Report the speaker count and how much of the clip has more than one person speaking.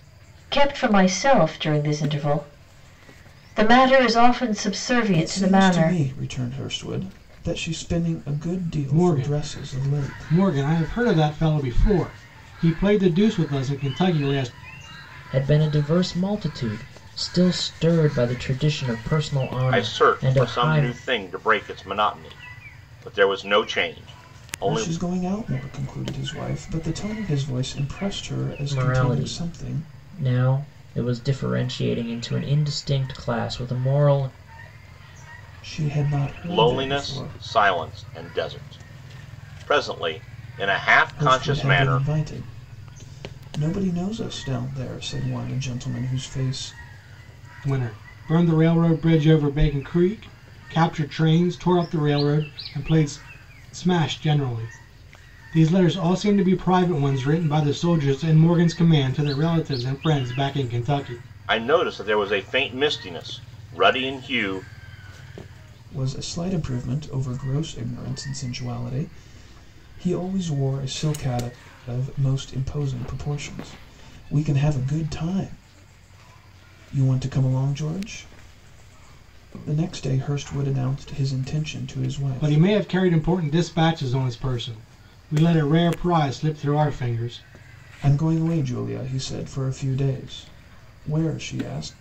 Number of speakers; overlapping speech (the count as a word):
five, about 8%